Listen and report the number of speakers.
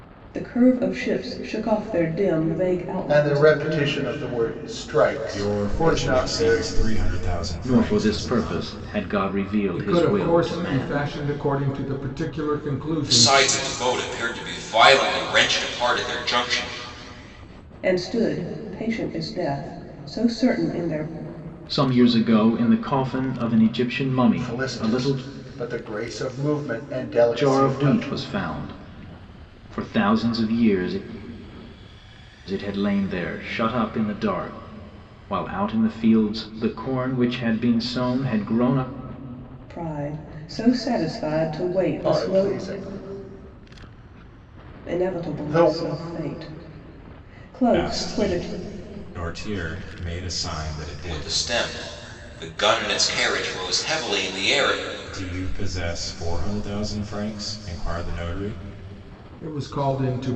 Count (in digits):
6